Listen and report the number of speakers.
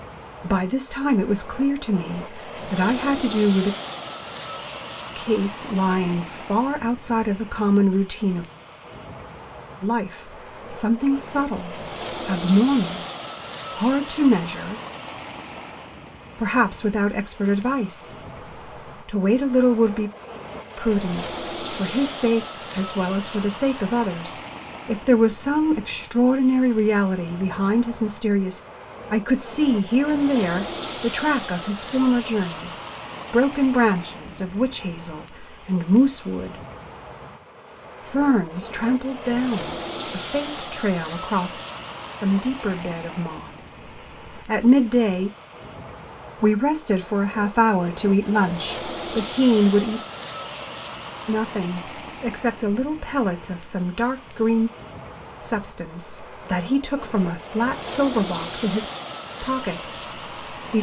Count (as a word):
one